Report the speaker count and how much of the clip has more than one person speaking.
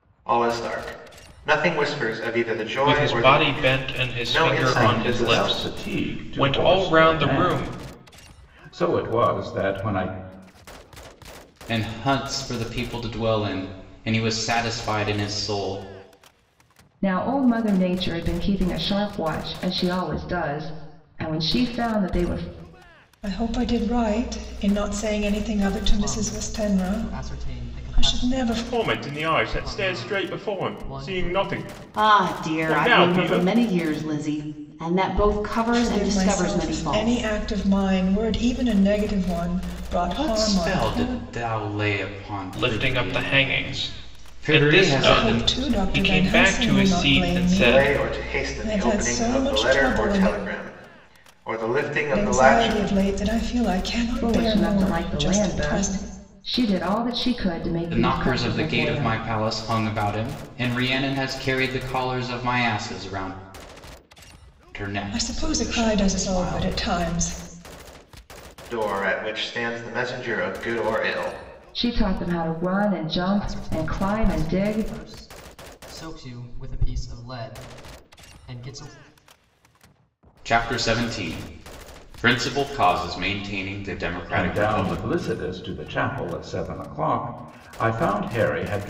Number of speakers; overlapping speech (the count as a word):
nine, about 35%